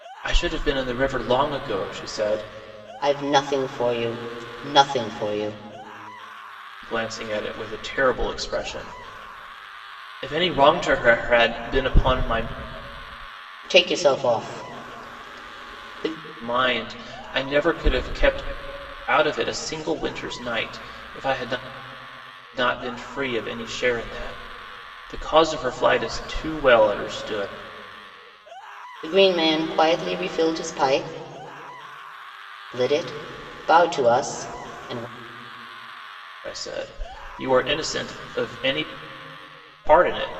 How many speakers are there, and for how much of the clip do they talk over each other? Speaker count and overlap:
2, no overlap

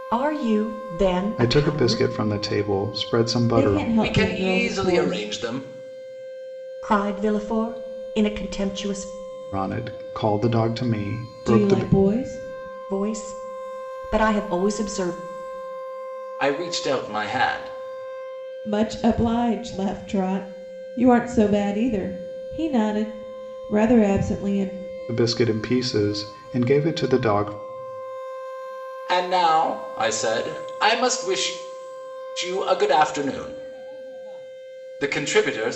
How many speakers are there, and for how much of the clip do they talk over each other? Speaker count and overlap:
4, about 8%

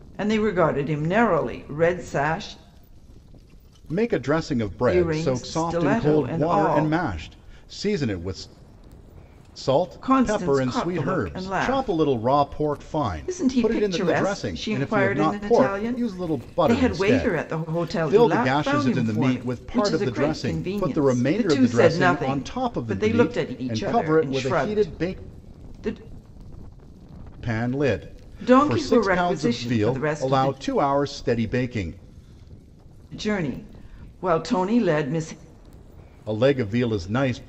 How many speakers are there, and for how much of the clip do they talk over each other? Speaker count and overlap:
2, about 49%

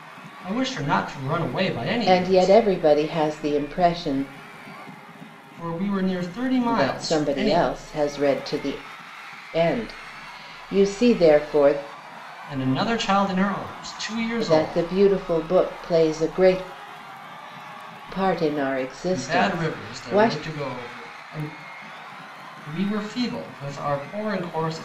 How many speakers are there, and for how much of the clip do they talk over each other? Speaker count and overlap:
2, about 13%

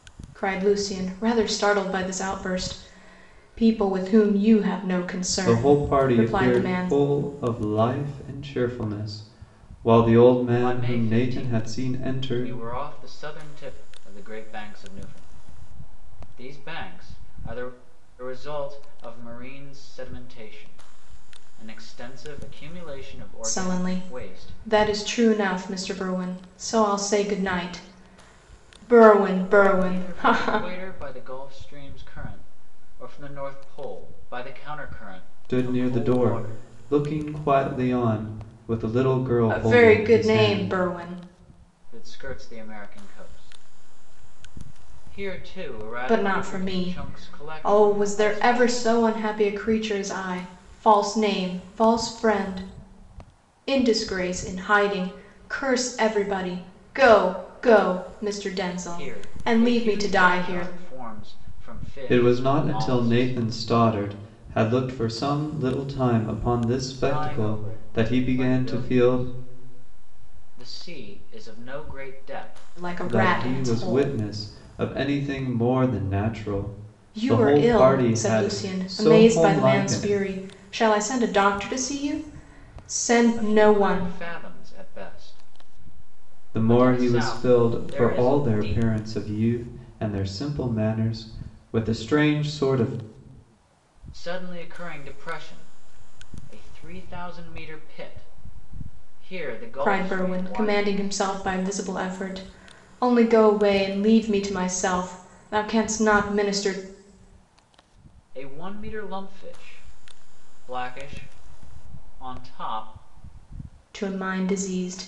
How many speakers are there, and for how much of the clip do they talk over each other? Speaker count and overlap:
3, about 23%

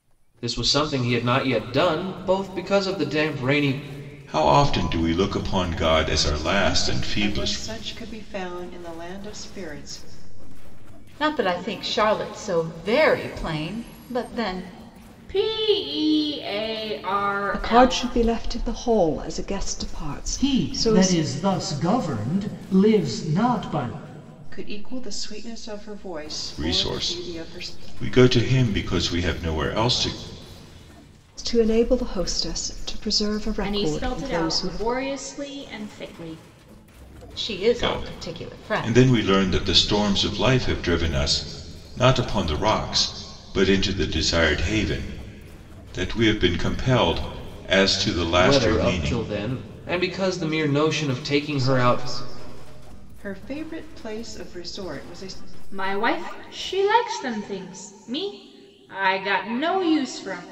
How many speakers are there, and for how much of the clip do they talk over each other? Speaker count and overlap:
7, about 13%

